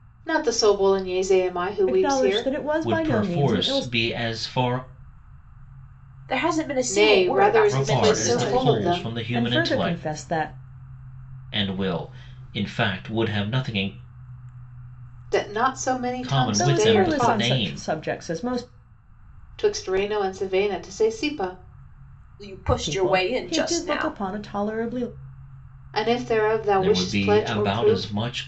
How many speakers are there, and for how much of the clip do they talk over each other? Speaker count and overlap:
4, about 34%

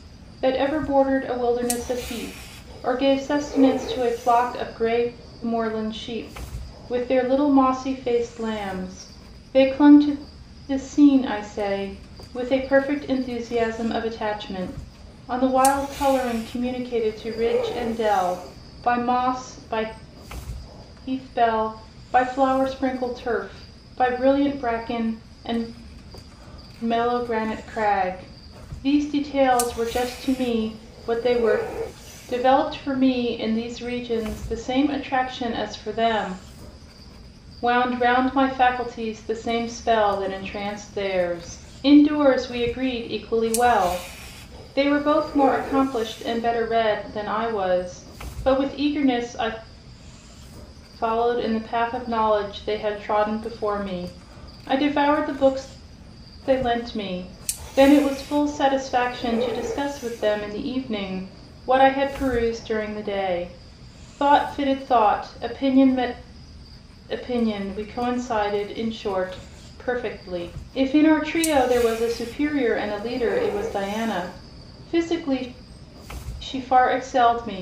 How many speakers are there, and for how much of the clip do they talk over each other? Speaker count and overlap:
1, no overlap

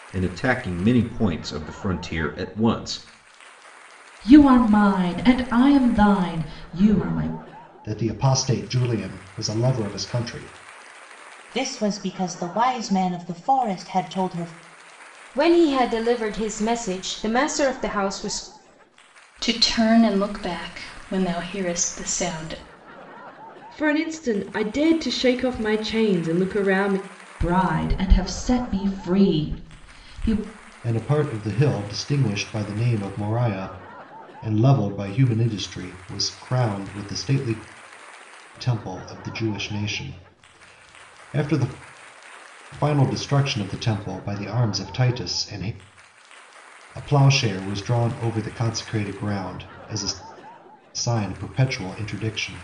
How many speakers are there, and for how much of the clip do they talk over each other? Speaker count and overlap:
7, no overlap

